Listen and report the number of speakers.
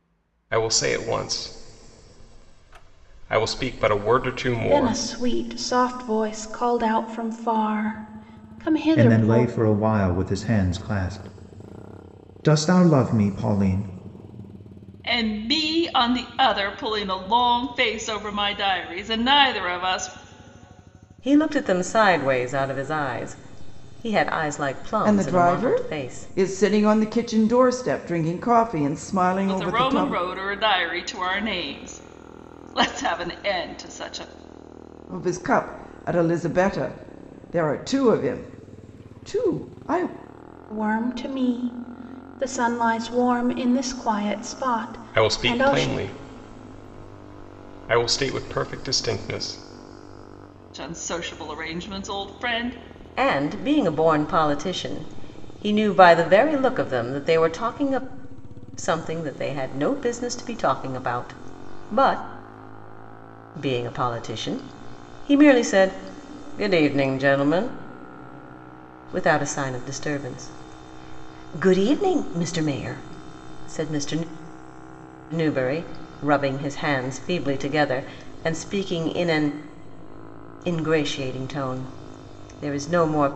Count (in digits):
6